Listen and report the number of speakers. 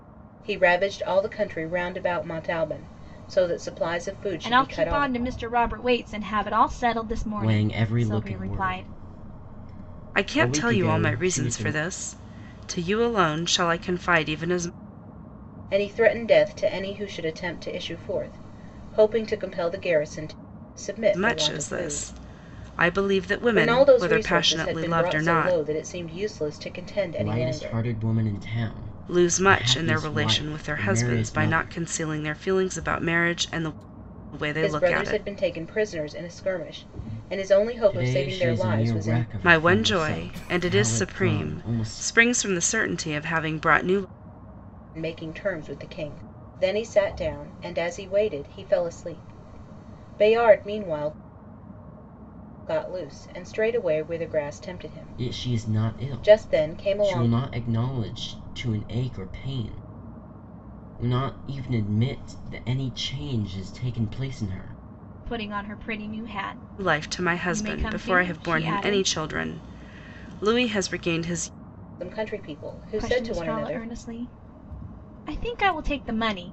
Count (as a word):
four